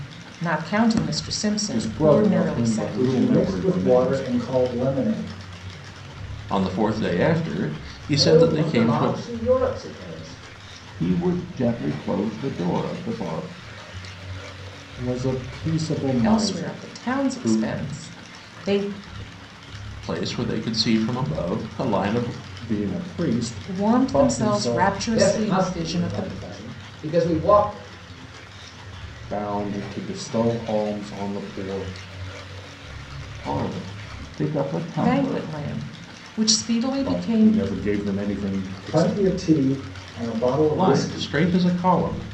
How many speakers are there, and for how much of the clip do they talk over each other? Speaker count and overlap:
6, about 23%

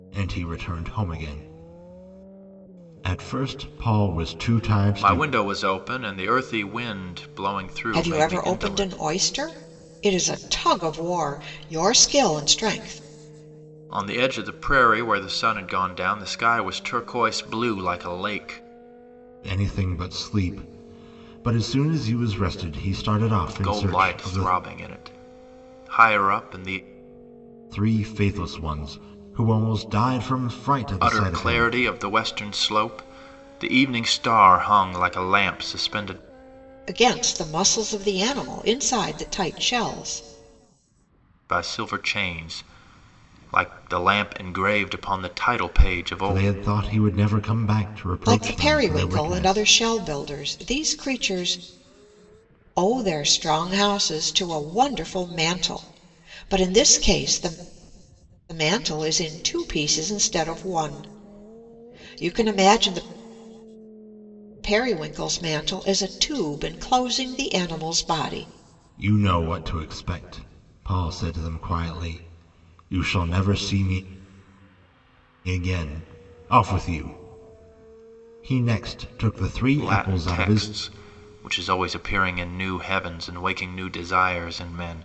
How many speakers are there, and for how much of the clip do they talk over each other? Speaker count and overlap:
3, about 7%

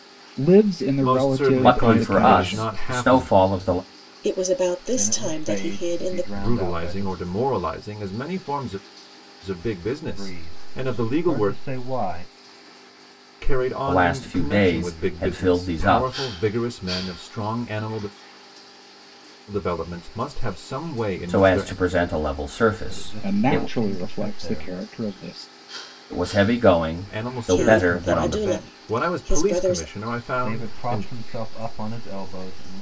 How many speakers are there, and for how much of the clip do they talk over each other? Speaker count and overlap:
5, about 44%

